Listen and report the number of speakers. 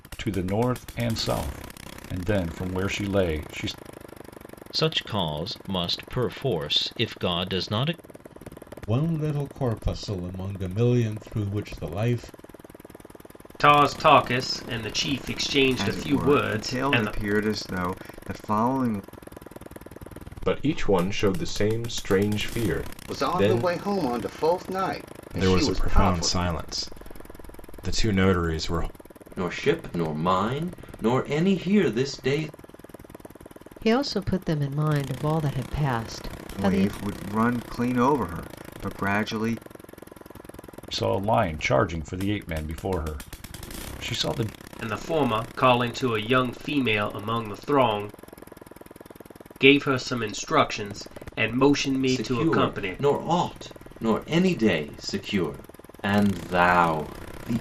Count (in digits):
10